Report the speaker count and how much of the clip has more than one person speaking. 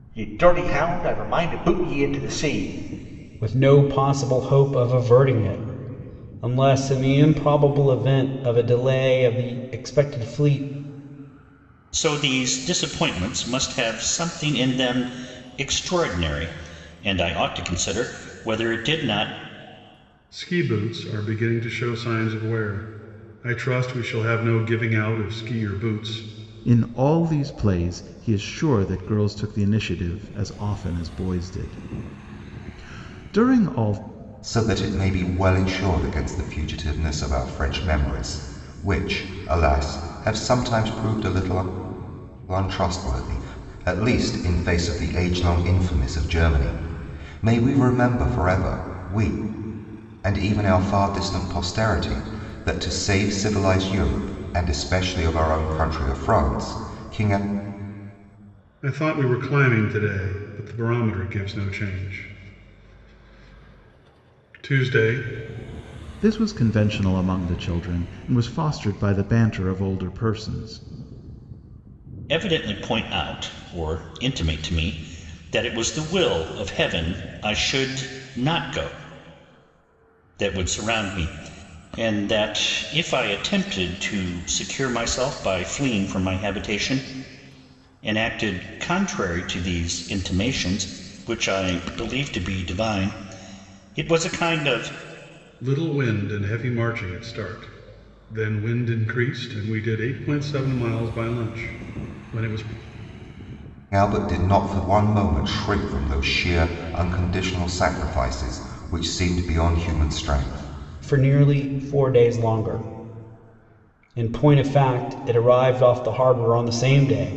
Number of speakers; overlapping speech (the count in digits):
6, no overlap